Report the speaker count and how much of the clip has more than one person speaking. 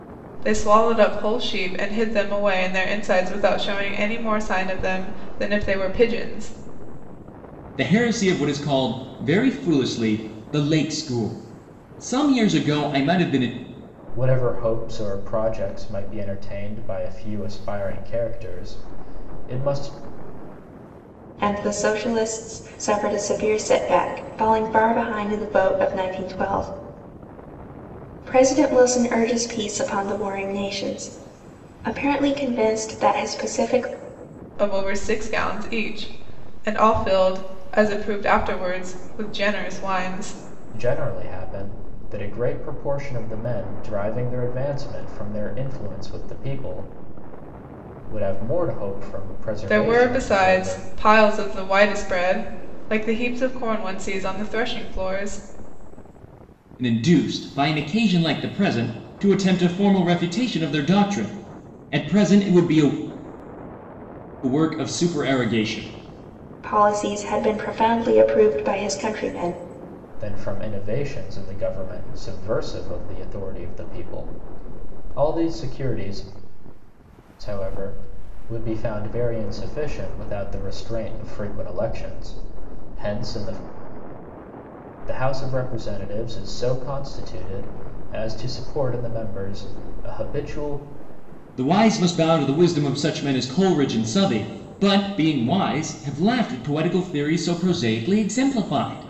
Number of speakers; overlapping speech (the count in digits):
4, about 1%